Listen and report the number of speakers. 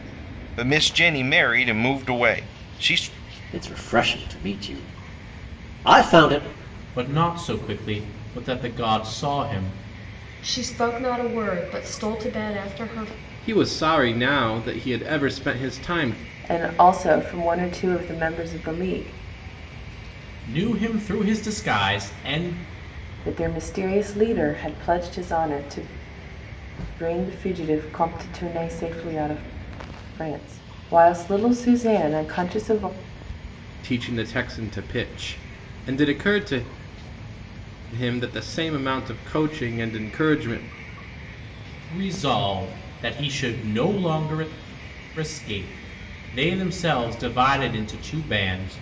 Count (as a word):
six